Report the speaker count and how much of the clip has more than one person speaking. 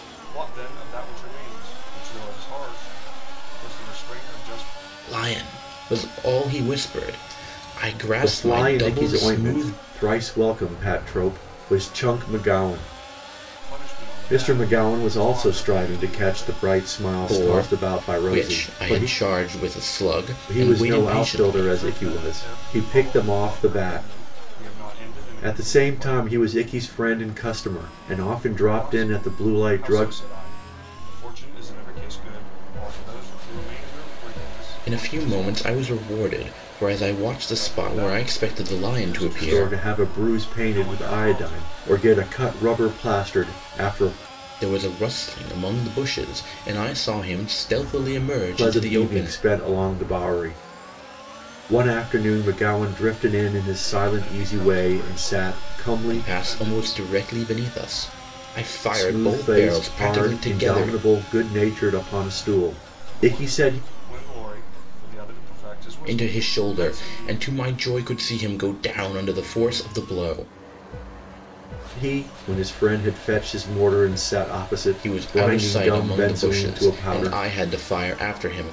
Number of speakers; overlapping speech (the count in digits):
3, about 36%